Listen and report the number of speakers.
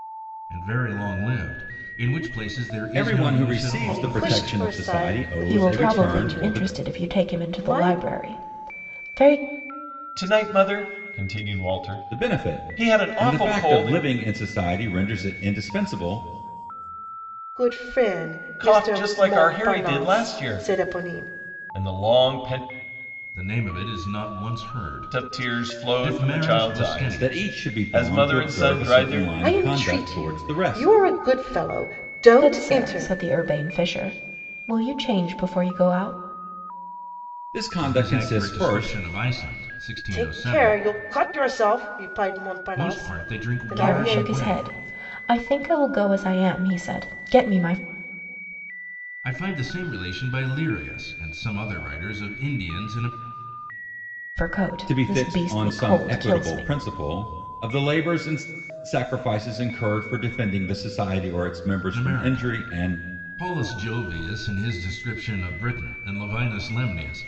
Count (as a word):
five